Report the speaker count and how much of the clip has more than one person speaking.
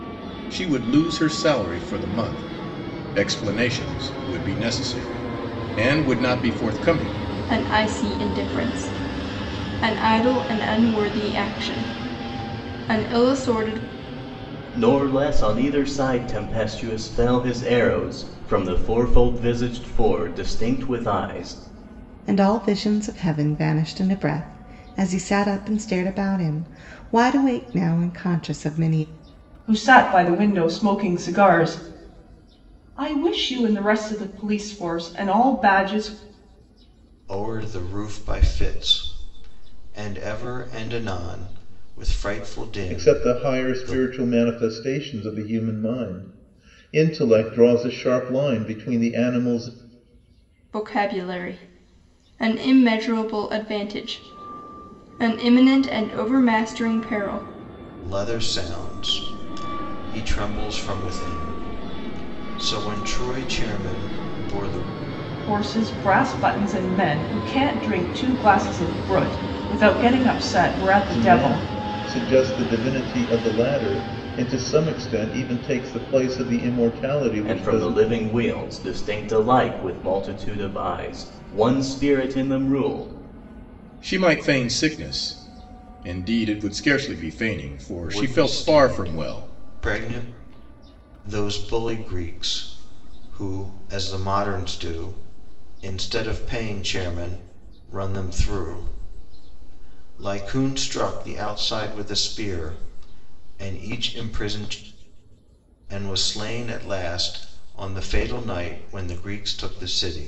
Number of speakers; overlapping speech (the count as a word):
seven, about 3%